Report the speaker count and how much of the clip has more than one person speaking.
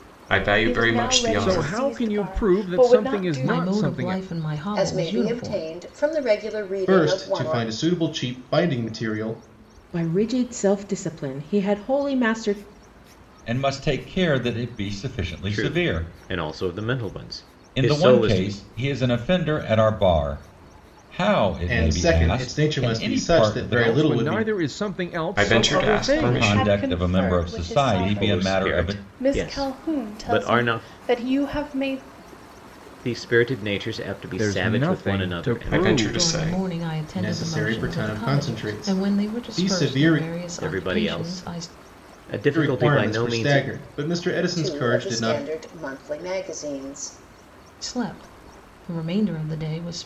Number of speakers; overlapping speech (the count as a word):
nine, about 47%